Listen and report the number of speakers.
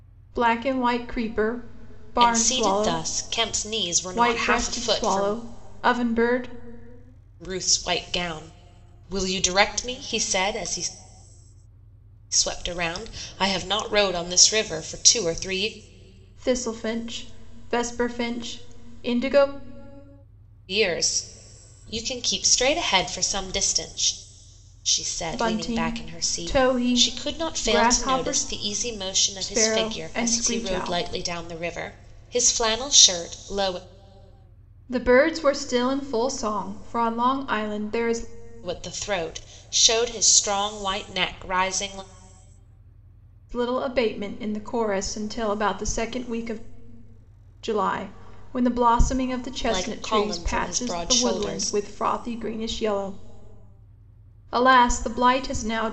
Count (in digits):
2